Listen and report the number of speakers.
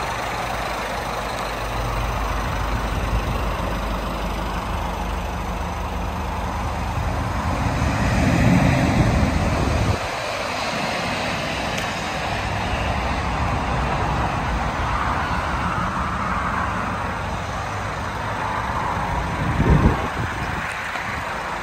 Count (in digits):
0